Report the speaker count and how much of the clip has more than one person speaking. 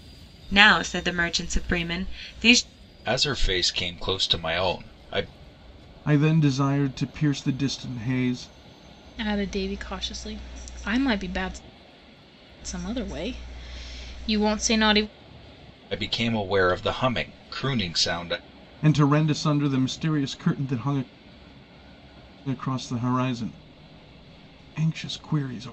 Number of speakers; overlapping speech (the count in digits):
4, no overlap